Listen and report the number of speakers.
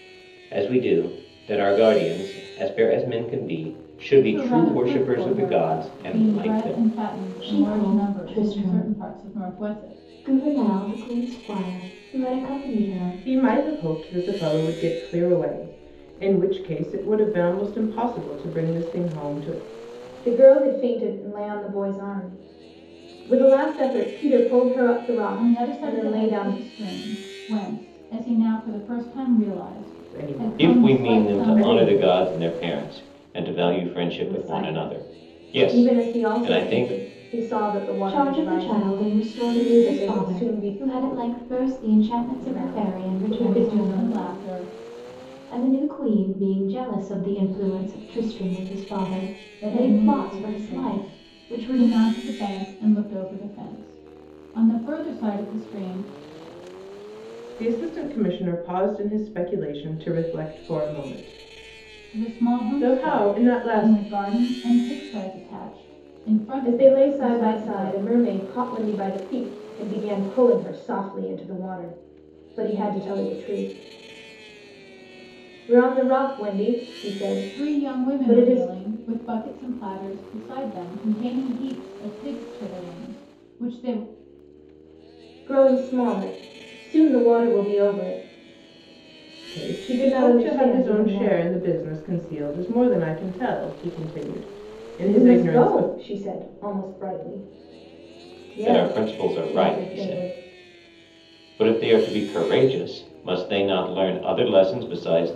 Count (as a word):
five